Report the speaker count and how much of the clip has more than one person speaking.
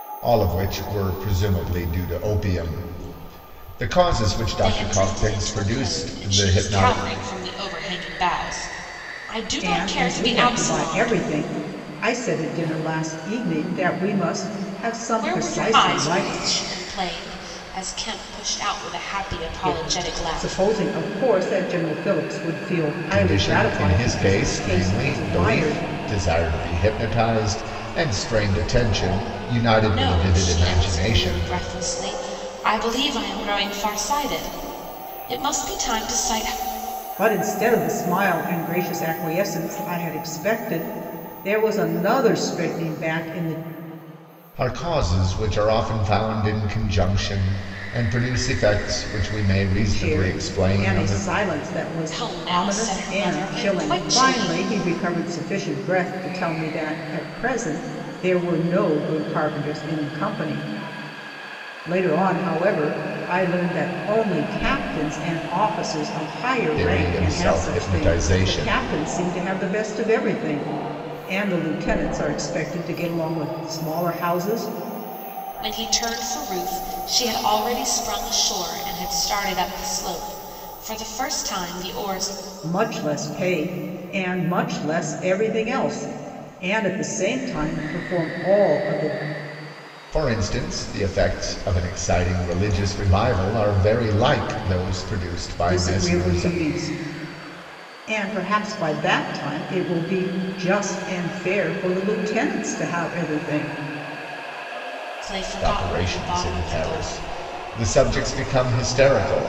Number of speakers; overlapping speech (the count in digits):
3, about 18%